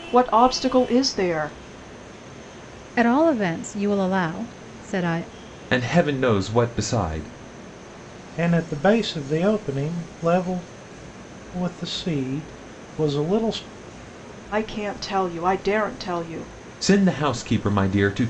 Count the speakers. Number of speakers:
4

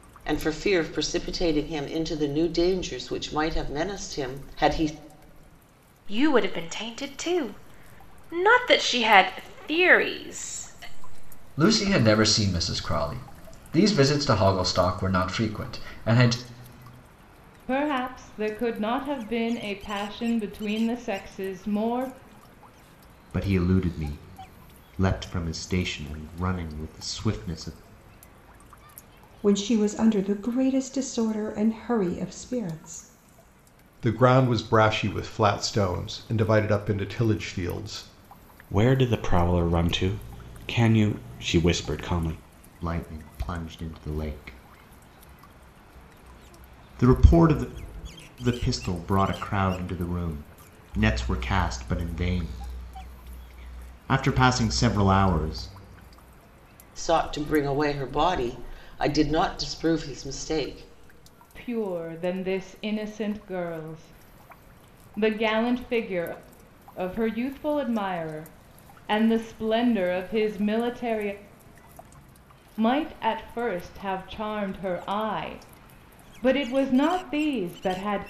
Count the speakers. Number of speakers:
8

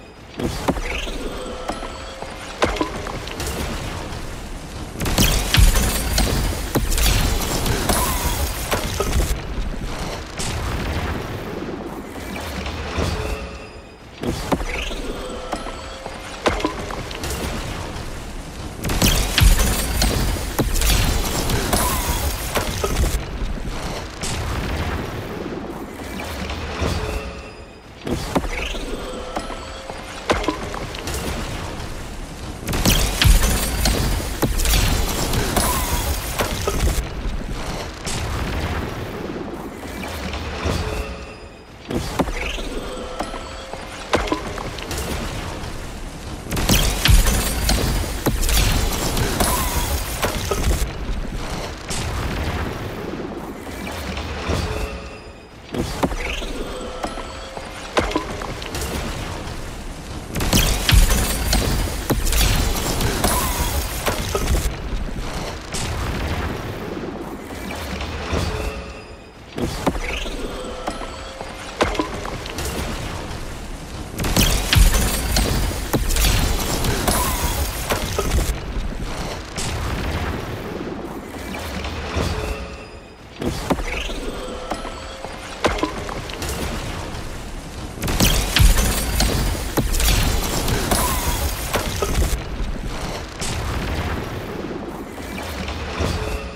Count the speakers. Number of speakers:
0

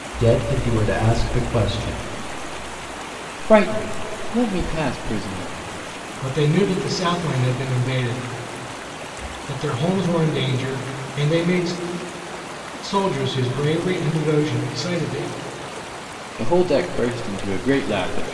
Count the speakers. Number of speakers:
3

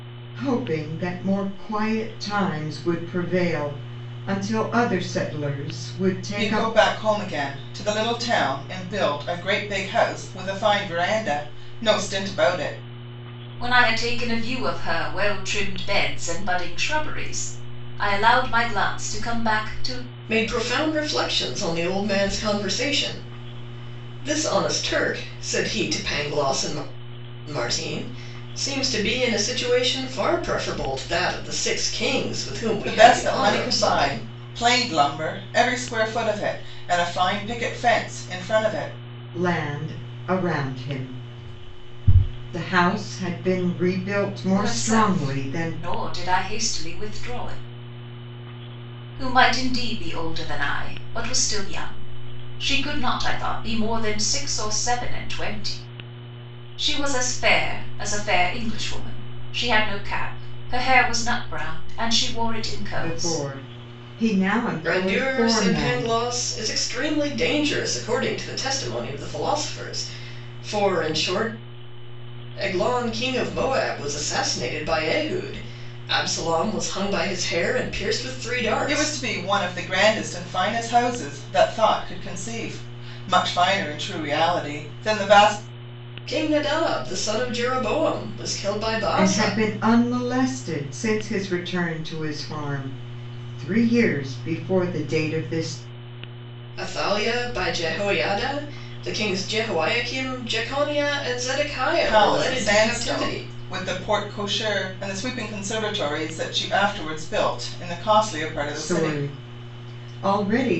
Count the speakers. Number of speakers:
4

